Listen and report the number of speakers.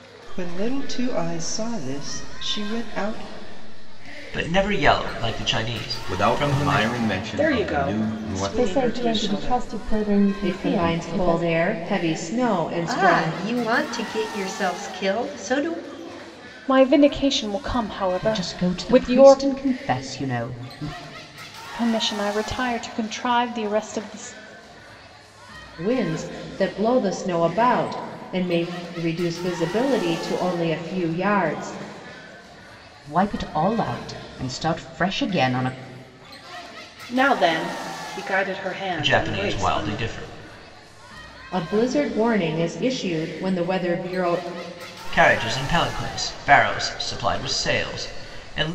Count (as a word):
nine